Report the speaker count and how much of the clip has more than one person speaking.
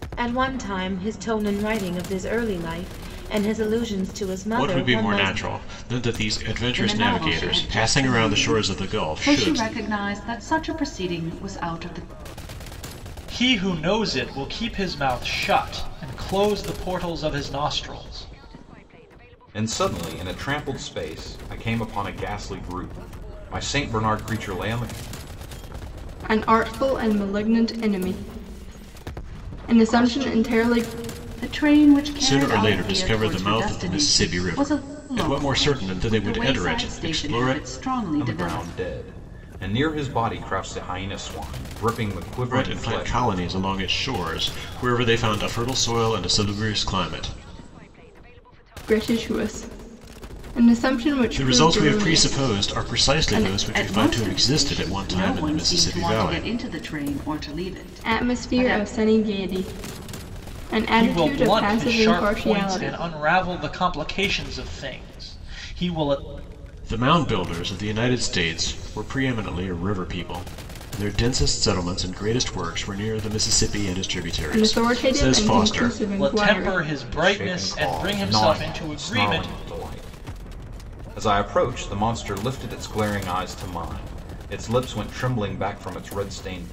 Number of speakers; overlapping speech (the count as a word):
six, about 28%